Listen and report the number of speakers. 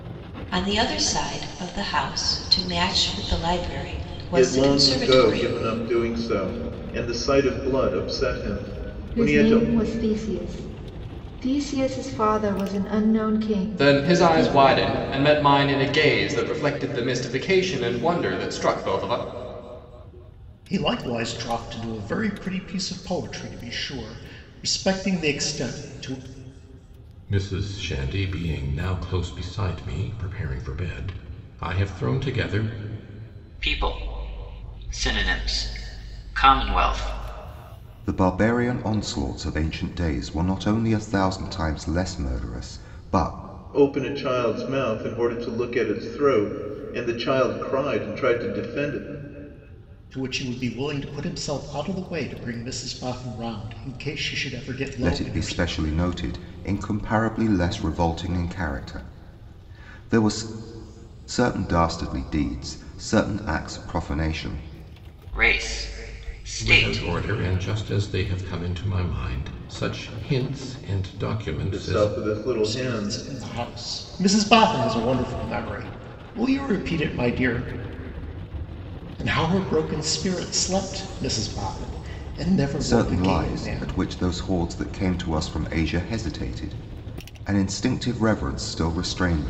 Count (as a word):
eight